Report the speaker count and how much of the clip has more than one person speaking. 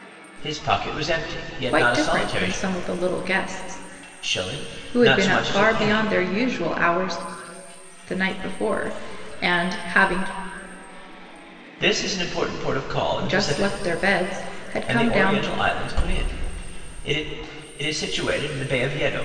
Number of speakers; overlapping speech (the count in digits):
2, about 18%